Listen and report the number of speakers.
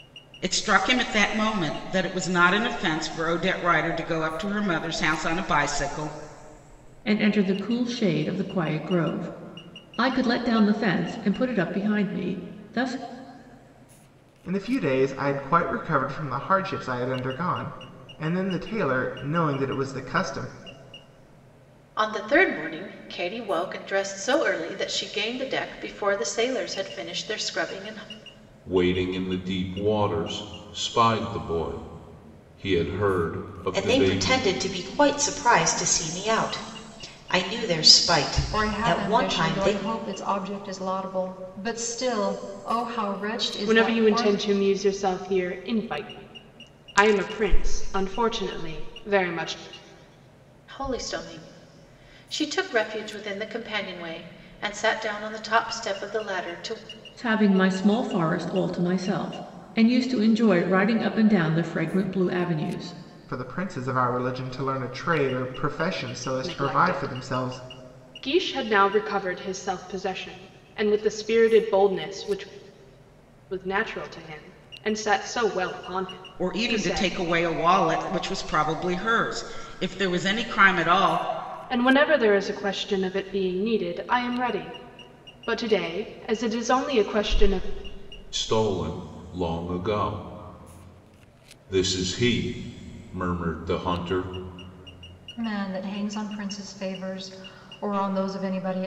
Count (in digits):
8